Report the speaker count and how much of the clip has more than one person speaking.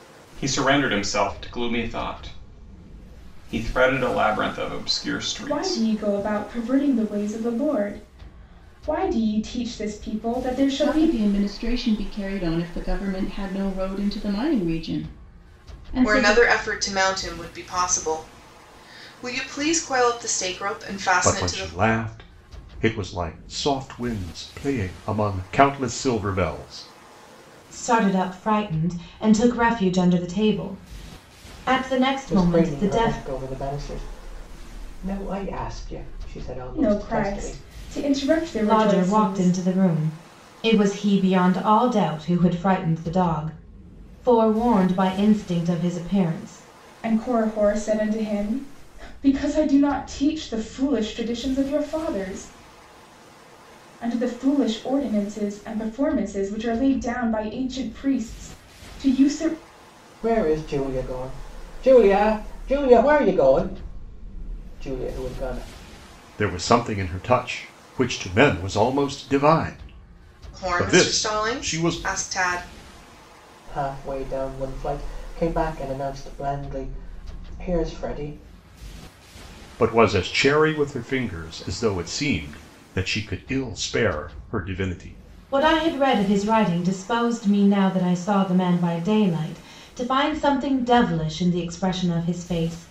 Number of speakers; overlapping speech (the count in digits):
7, about 7%